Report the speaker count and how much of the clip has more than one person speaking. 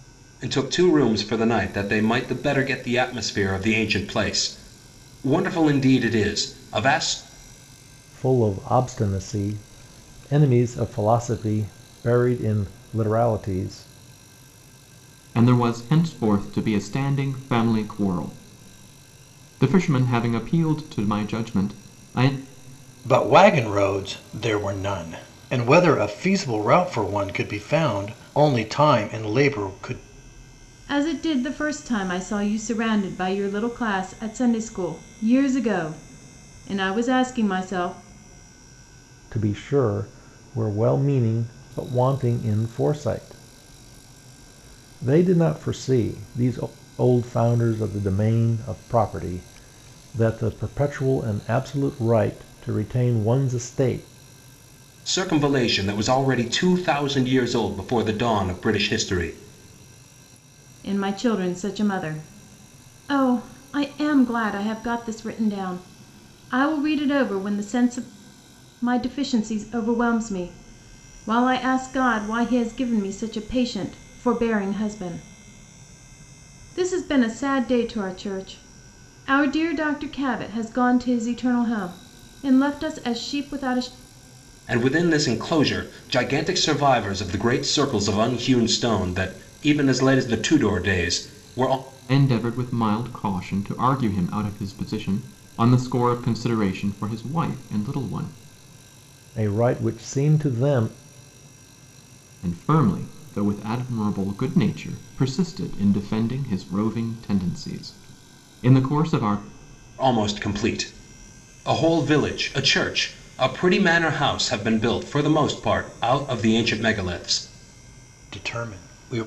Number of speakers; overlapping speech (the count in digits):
5, no overlap